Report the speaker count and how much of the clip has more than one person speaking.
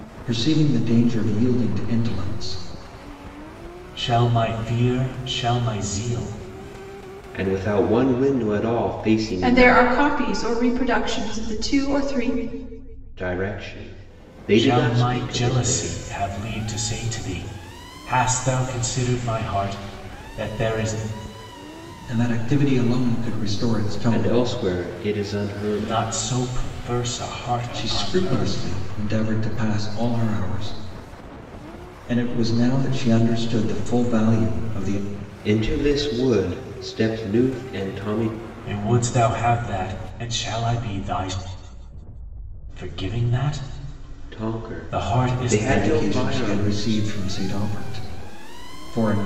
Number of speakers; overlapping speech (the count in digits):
4, about 13%